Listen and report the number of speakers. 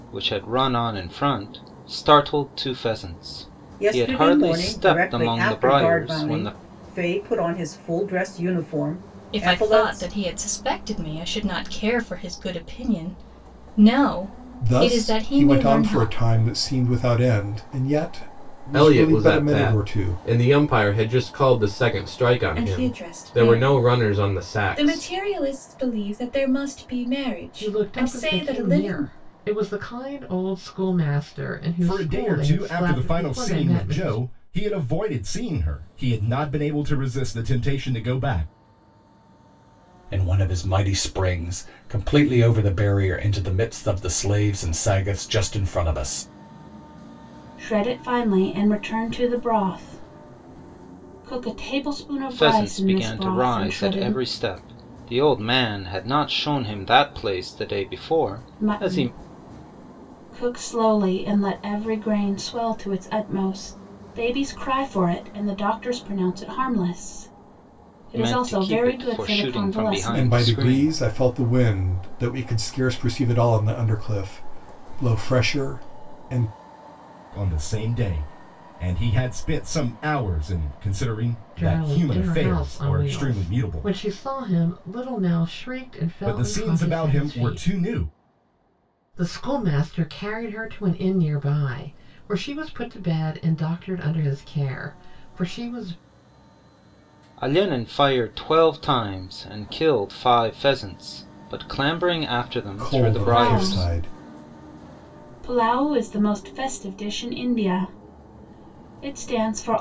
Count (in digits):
10